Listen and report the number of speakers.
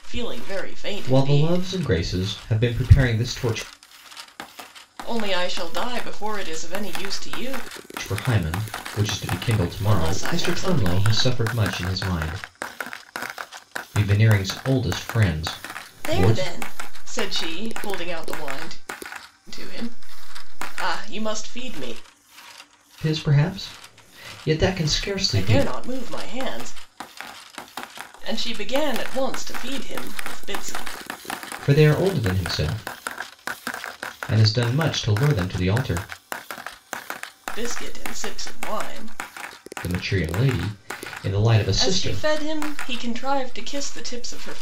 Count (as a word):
two